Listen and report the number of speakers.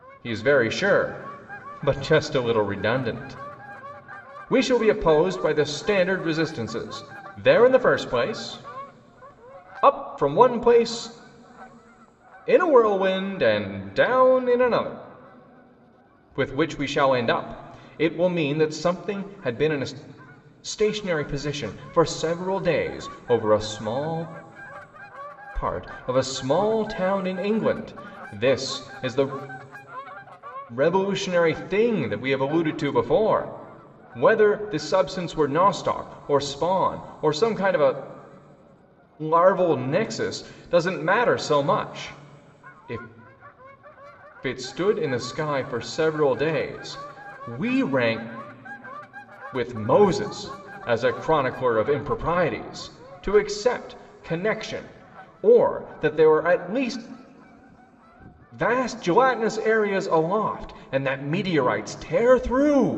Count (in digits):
1